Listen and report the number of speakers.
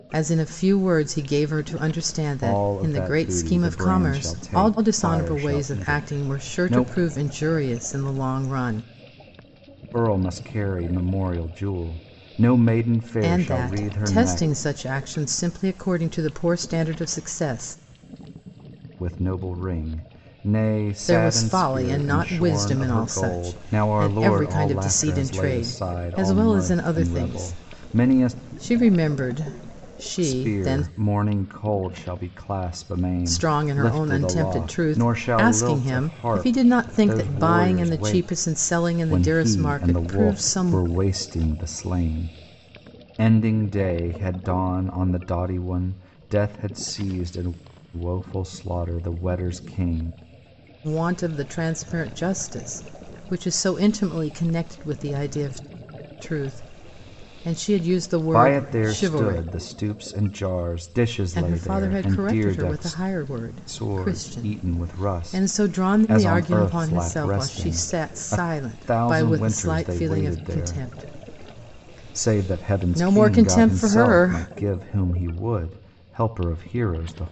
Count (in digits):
2